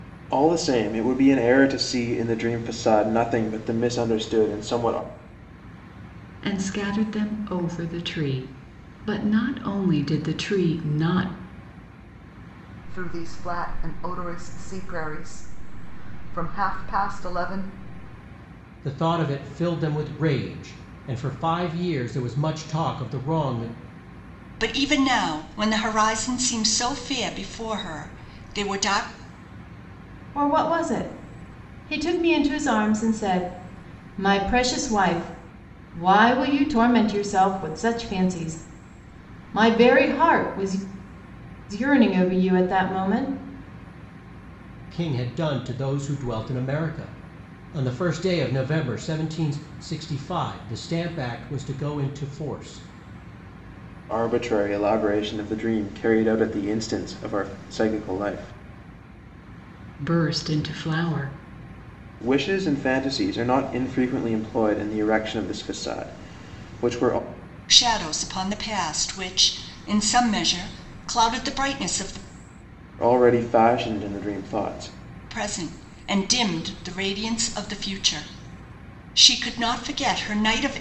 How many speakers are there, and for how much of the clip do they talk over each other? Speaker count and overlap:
6, no overlap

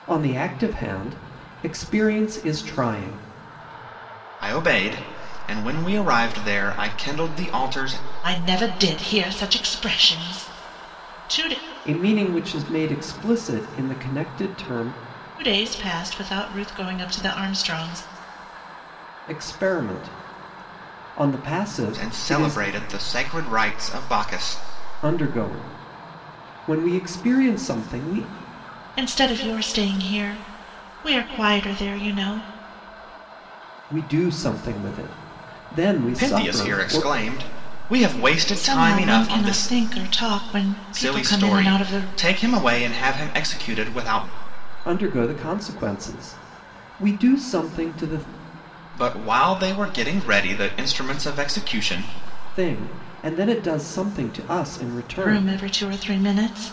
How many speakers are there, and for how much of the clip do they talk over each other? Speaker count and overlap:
3, about 8%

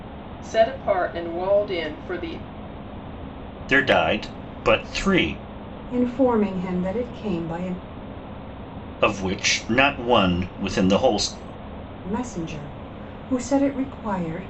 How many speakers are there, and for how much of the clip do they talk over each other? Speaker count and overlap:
3, no overlap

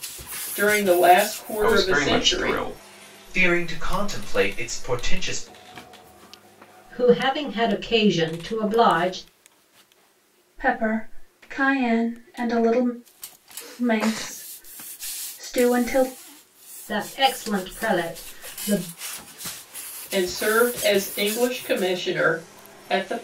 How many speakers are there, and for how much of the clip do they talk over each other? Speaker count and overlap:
5, about 4%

